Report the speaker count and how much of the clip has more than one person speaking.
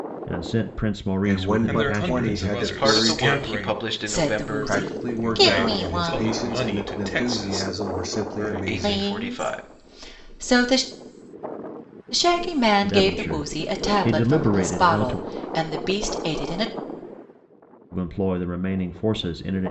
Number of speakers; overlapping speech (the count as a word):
five, about 50%